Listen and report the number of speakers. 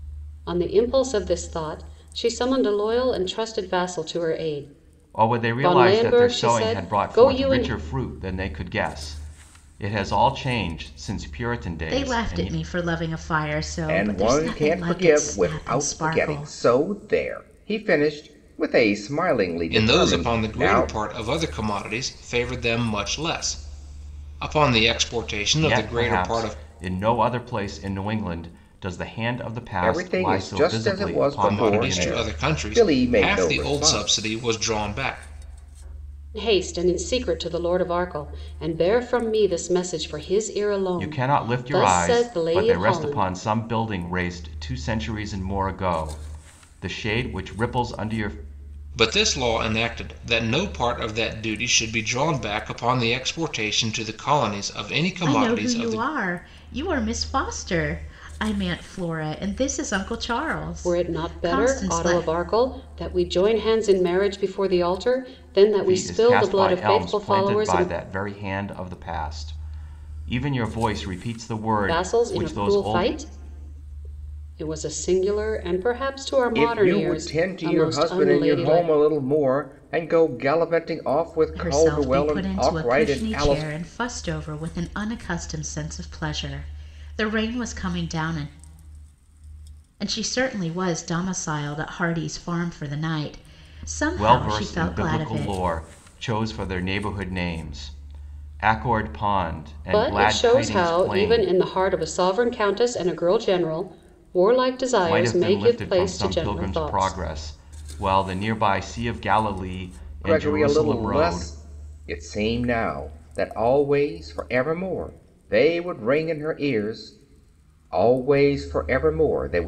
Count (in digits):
5